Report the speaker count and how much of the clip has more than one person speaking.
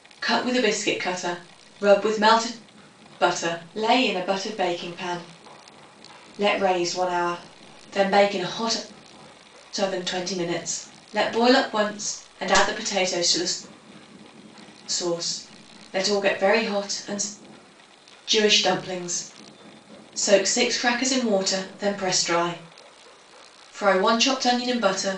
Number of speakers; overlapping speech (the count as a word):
one, no overlap